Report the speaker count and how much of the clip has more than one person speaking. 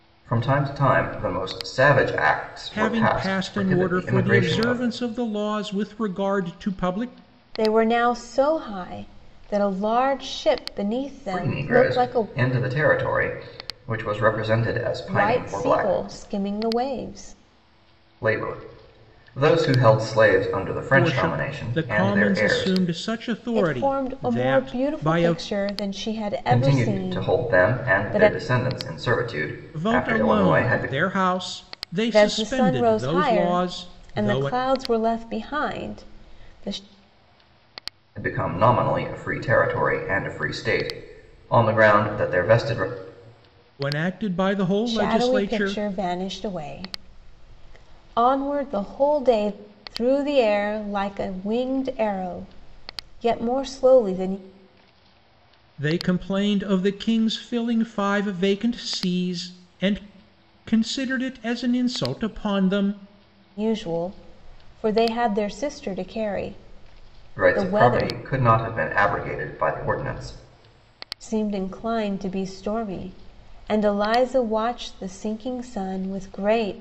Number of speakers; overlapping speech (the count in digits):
3, about 20%